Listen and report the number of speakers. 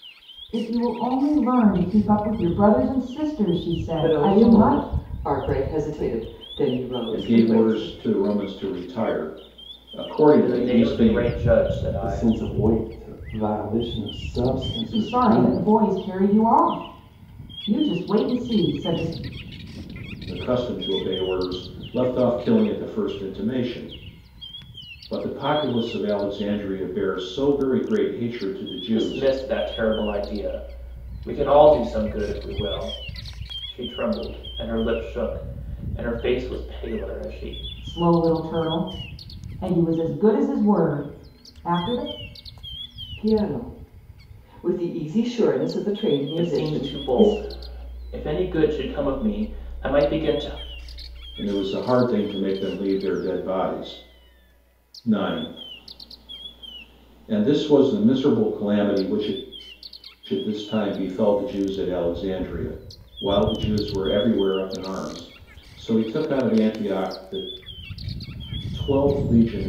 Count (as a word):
five